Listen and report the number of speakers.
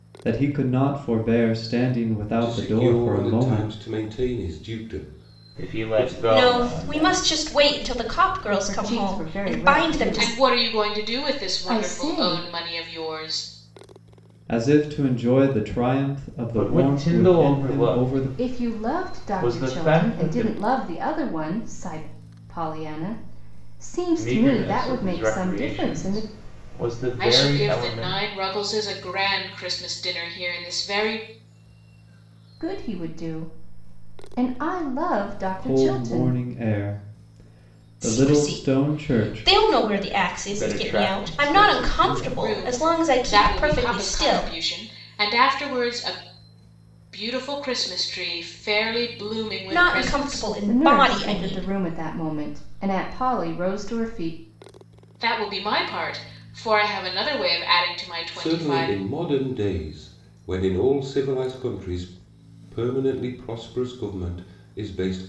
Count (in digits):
6